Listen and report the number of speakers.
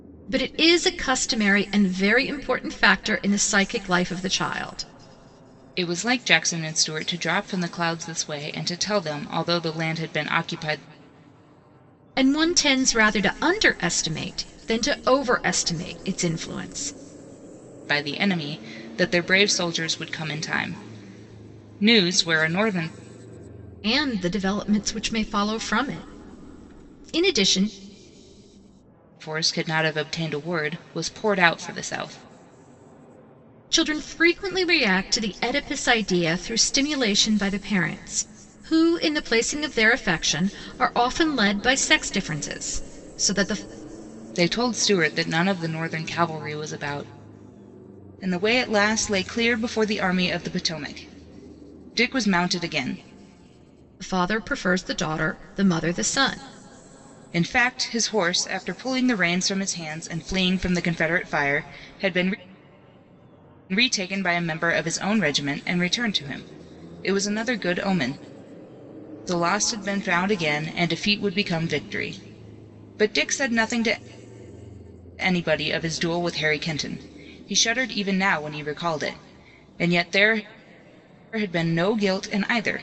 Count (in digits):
2